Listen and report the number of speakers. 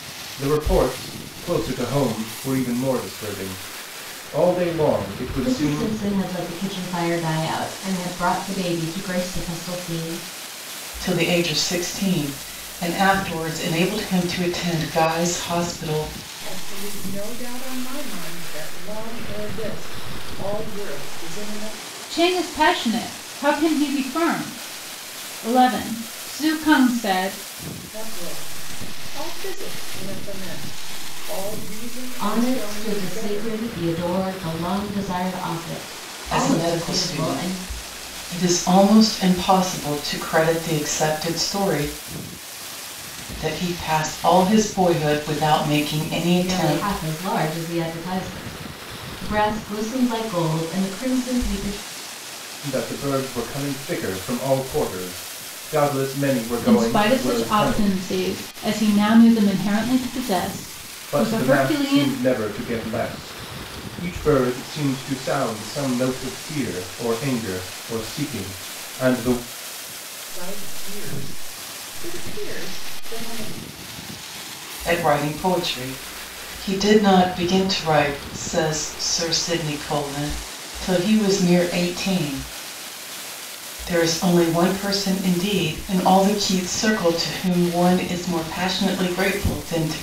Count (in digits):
5